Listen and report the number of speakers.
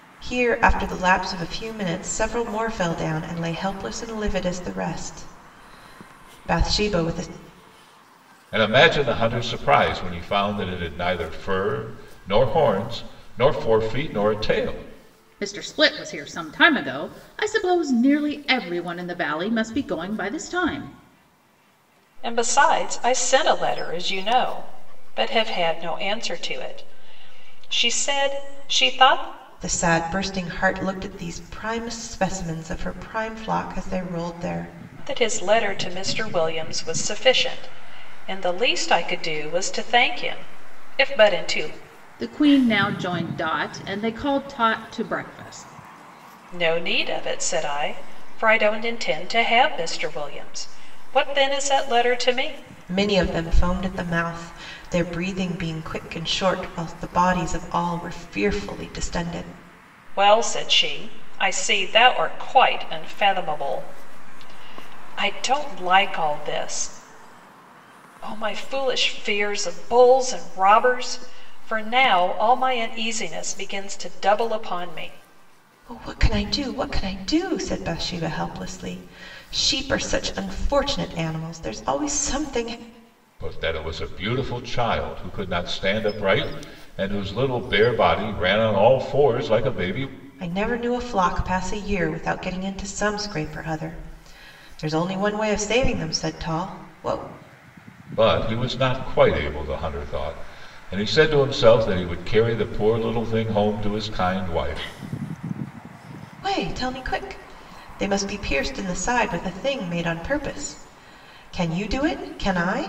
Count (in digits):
4